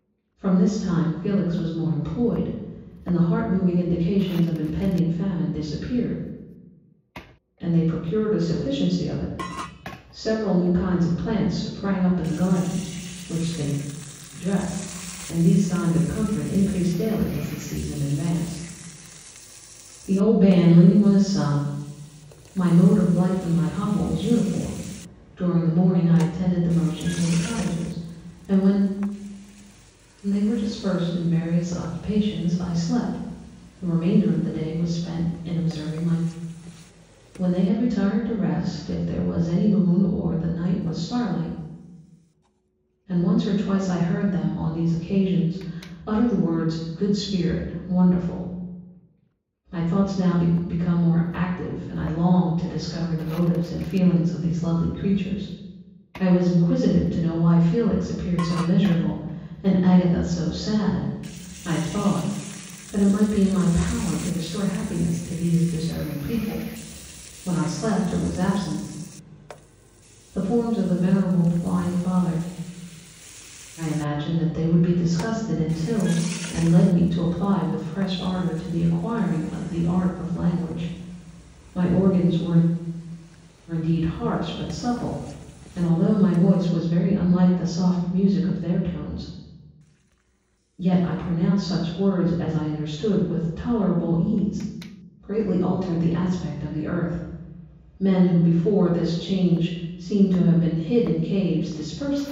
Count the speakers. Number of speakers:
one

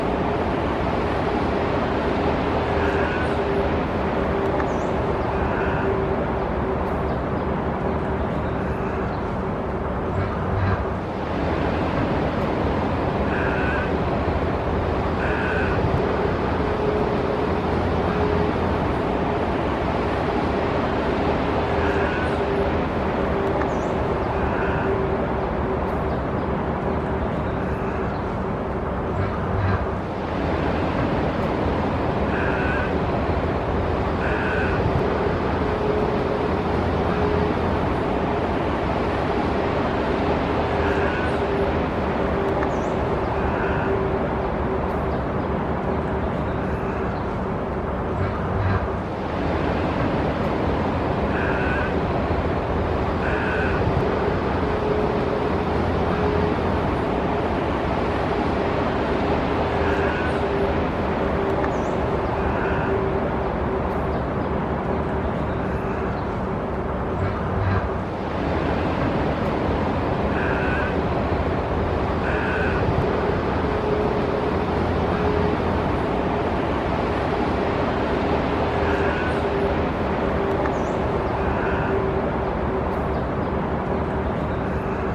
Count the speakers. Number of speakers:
zero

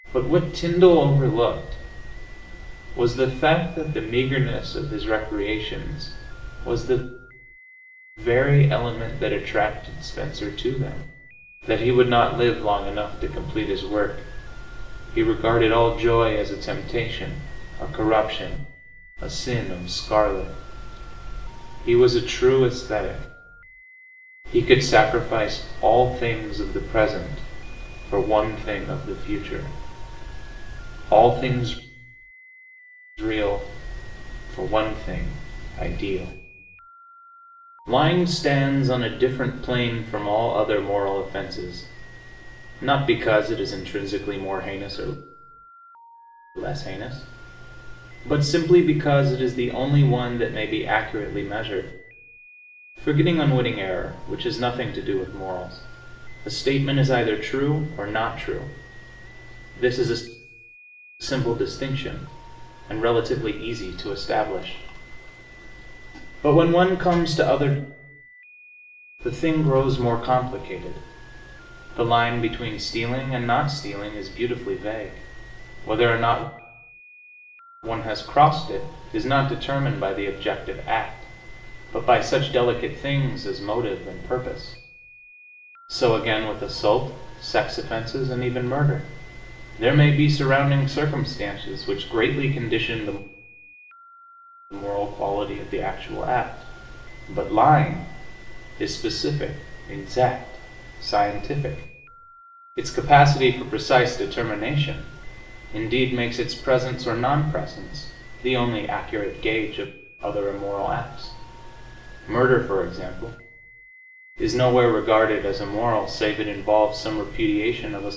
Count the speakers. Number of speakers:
one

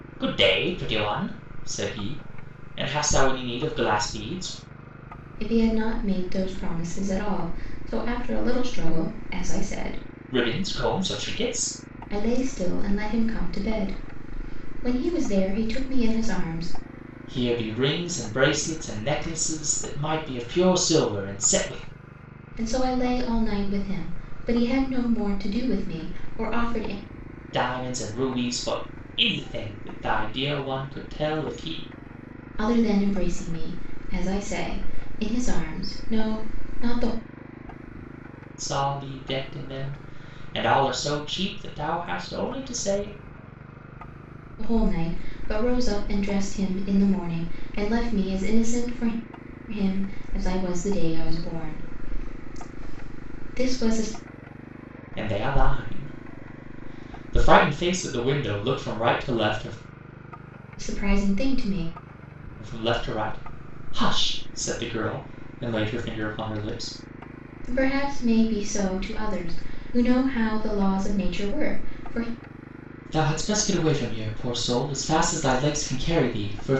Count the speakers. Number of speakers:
two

